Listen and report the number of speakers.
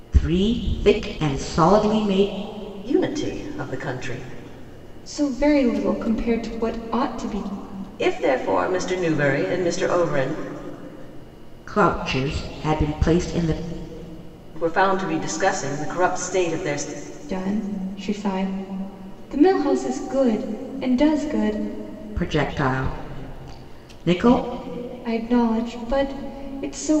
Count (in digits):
3